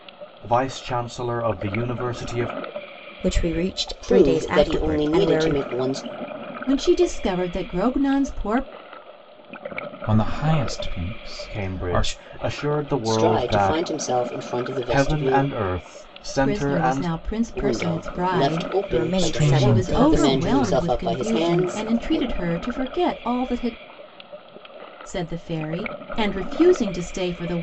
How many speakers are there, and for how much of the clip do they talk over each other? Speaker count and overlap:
5, about 34%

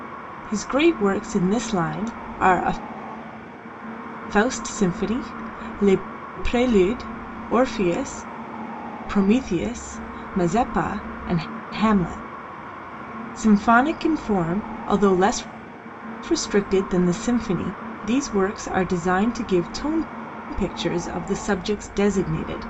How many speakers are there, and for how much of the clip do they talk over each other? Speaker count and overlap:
1, no overlap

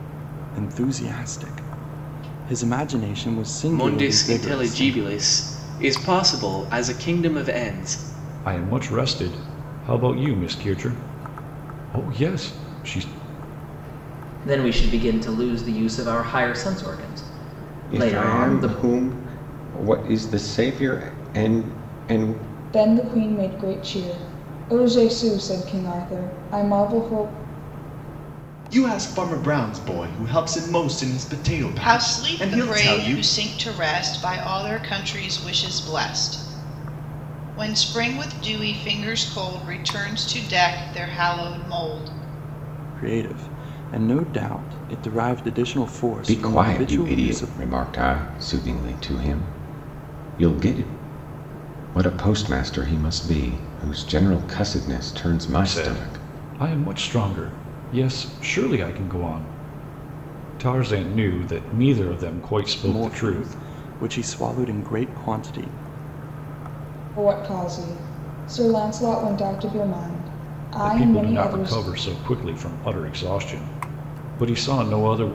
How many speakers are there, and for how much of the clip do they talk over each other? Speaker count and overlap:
8, about 10%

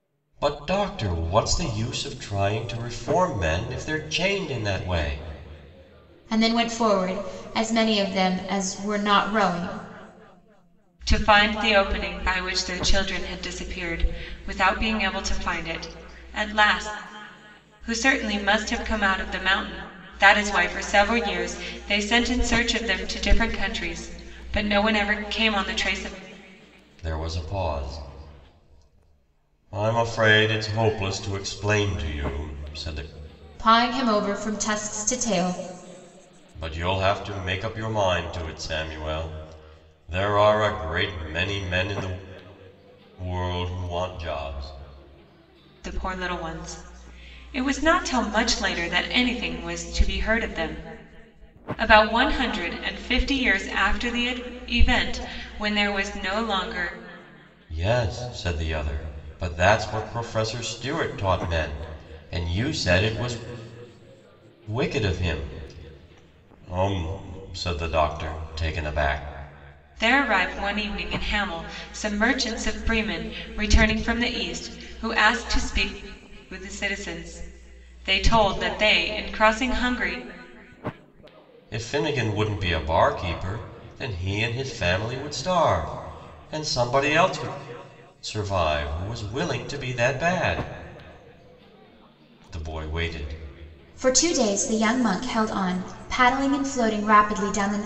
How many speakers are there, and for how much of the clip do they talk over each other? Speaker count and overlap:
3, no overlap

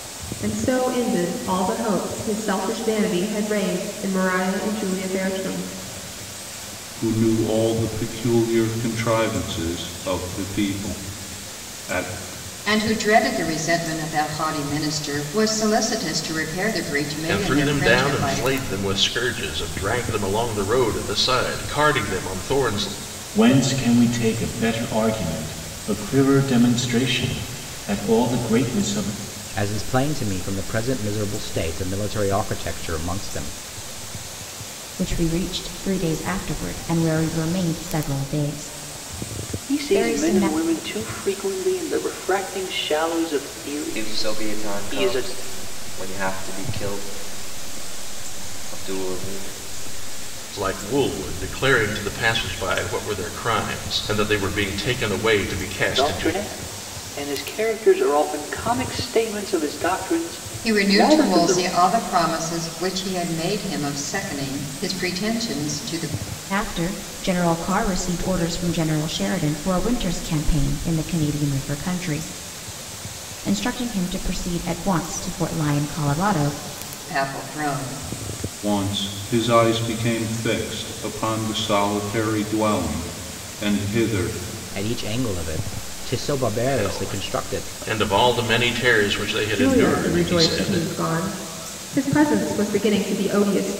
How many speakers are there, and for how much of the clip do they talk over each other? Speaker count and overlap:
9, about 8%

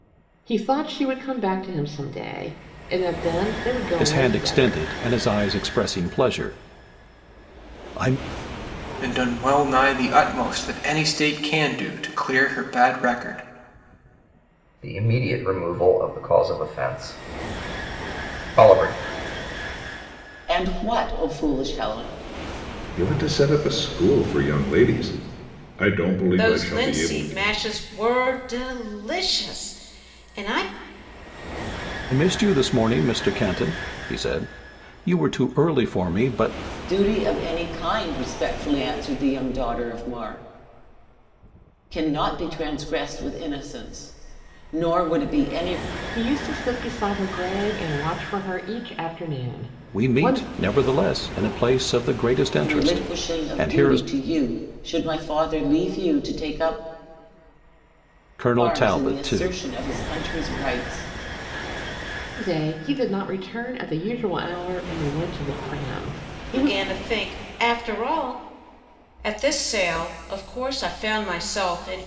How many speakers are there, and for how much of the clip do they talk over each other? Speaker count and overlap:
7, about 7%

